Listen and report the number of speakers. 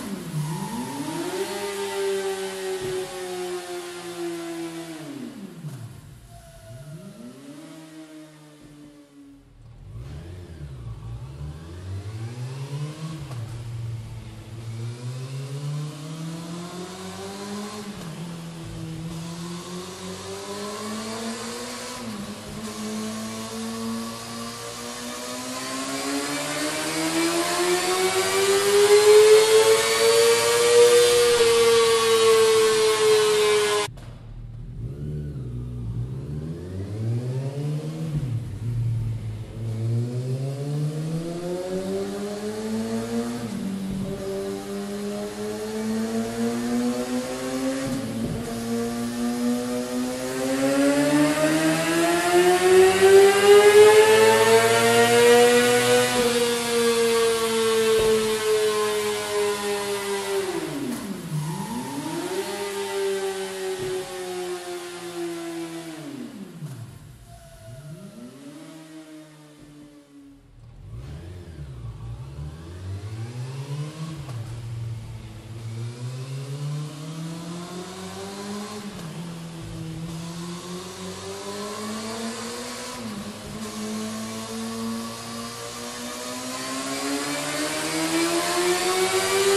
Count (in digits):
0